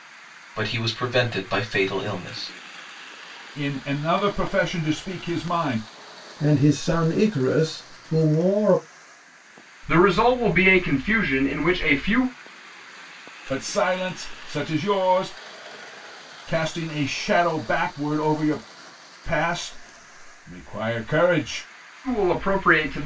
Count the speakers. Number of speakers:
4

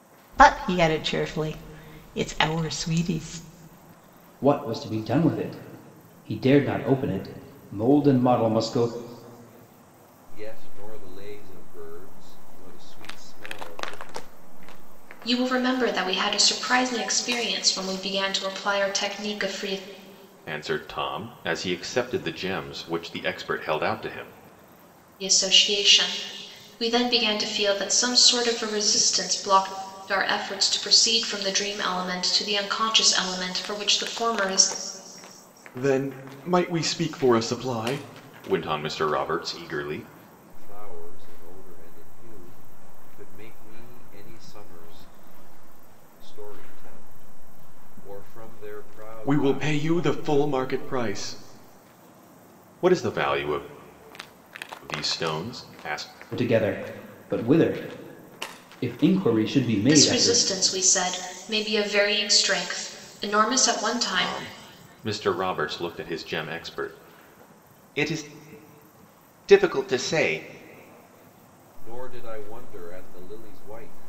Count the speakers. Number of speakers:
5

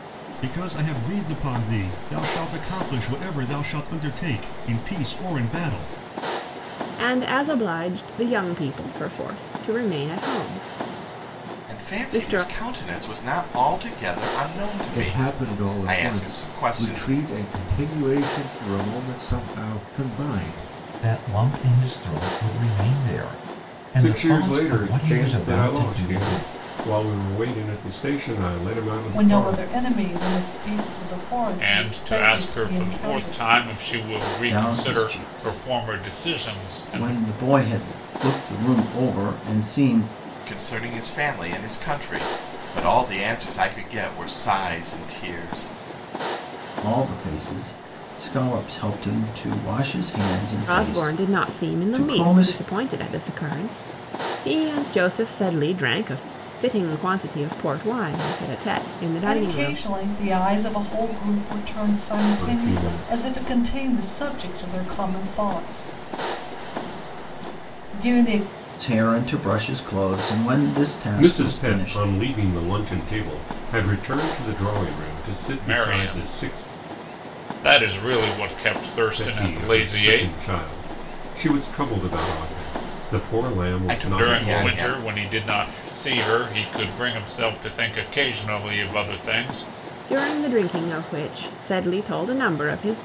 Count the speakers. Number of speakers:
9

